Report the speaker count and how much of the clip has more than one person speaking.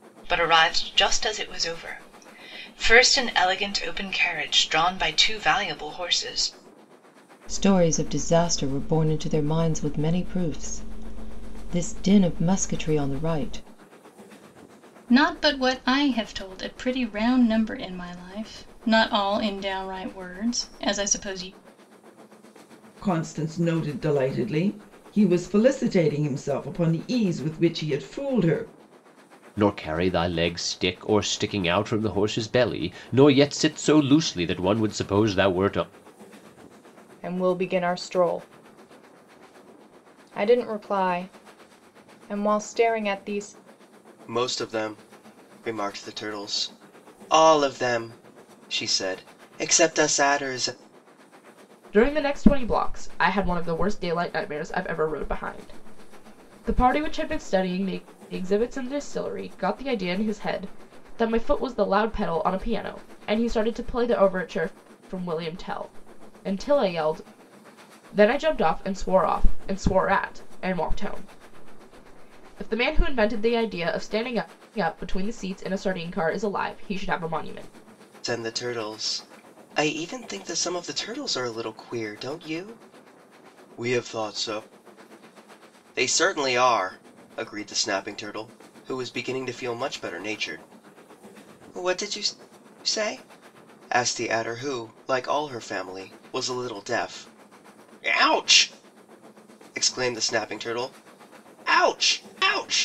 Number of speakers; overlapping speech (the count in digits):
8, no overlap